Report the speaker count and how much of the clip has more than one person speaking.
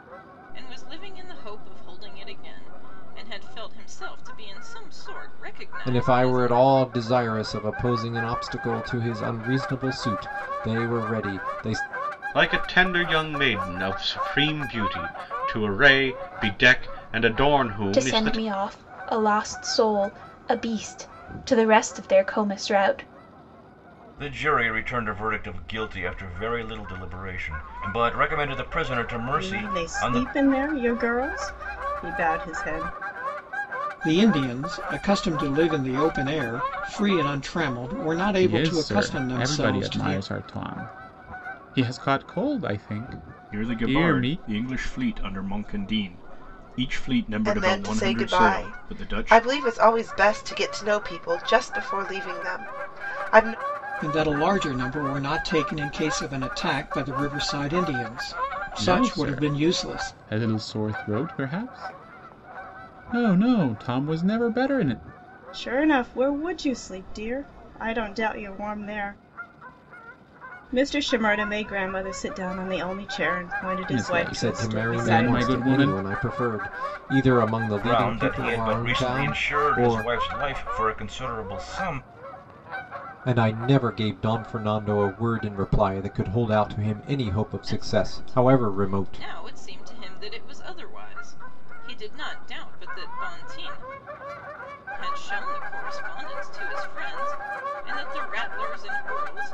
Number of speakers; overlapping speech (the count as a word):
ten, about 15%